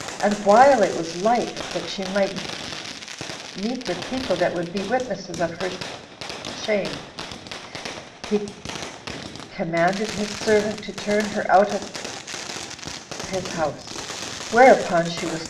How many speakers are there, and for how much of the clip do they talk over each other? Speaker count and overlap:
1, no overlap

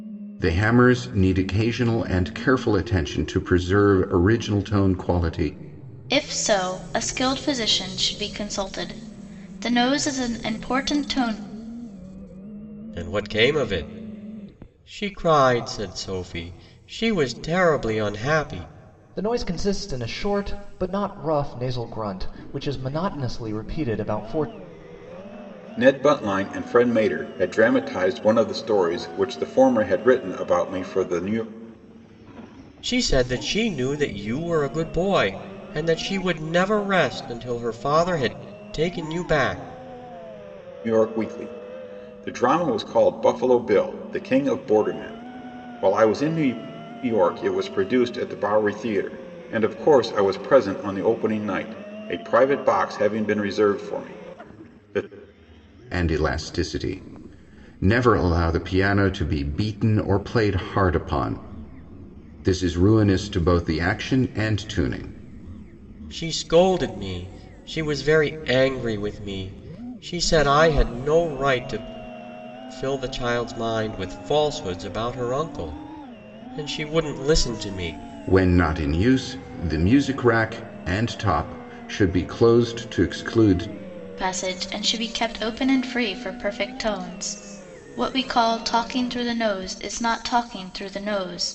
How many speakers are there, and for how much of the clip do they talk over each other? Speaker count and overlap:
5, no overlap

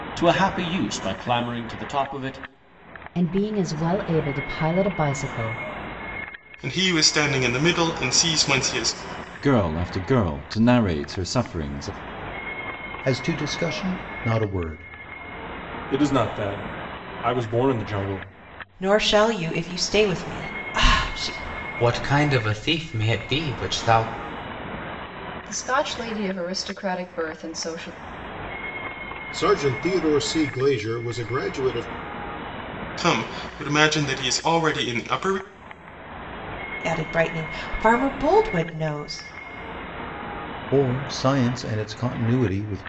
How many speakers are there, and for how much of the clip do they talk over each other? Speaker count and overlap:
10, no overlap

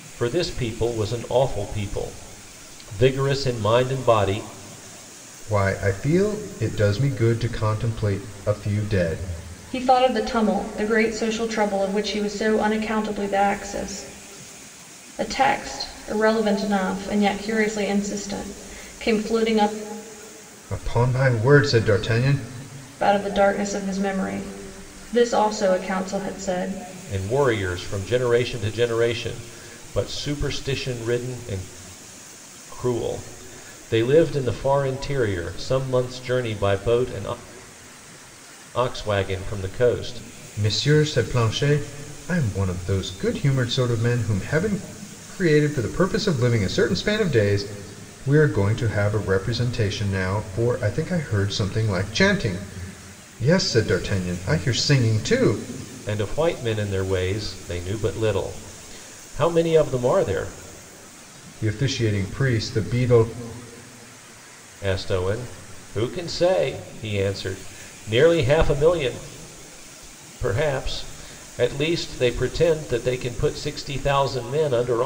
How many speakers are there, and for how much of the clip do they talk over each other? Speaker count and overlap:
3, no overlap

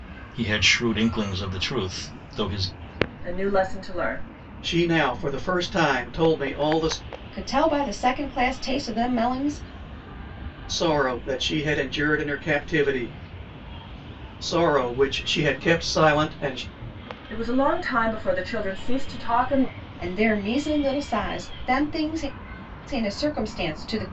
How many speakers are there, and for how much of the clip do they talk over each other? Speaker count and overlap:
4, no overlap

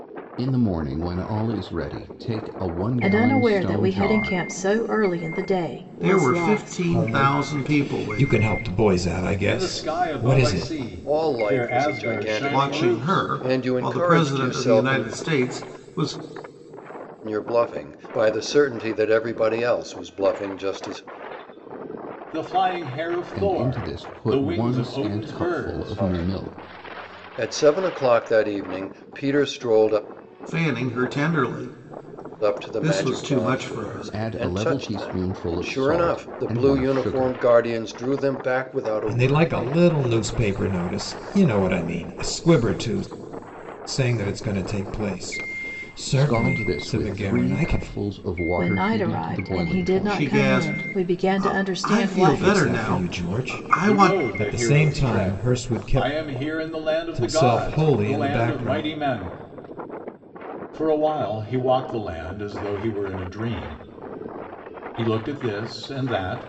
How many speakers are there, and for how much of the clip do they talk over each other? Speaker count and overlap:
6, about 46%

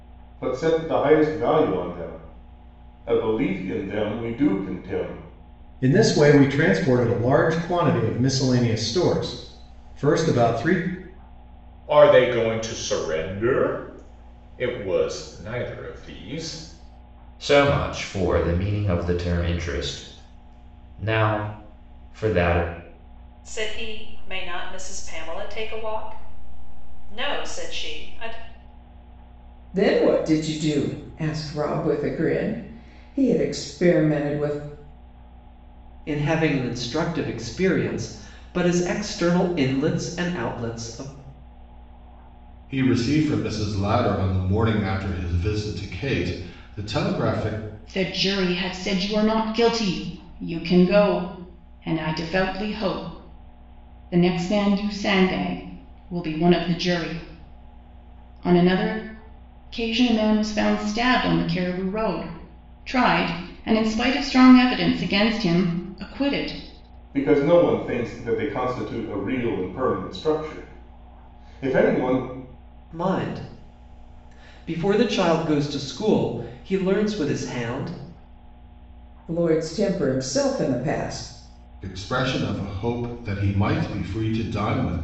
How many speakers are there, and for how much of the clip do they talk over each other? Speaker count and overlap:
9, no overlap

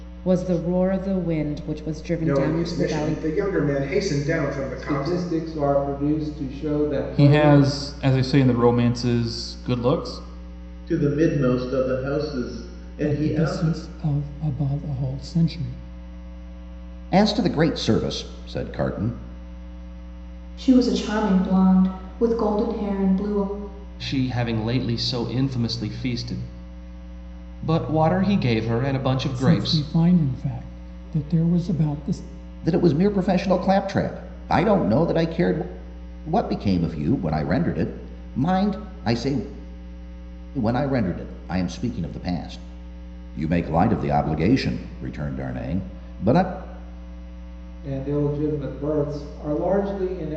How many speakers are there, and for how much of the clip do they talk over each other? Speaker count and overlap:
9, about 7%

